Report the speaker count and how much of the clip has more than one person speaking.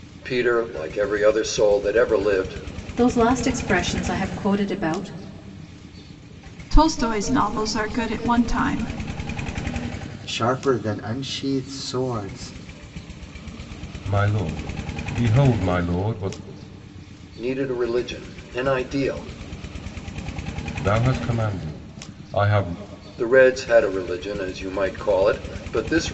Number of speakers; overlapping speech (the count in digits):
5, no overlap